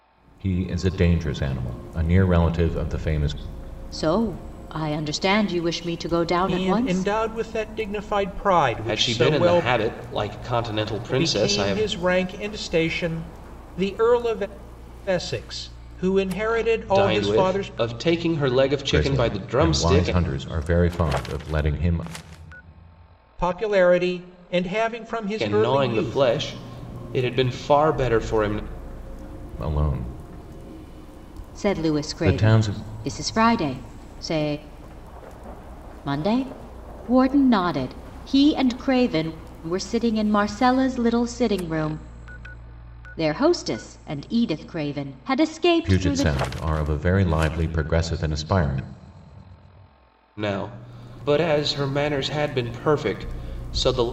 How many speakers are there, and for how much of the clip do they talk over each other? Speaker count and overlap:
4, about 14%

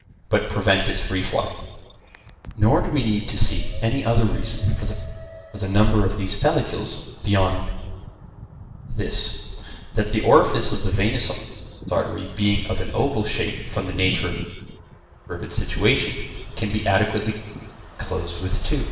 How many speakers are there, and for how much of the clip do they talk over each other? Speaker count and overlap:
1, no overlap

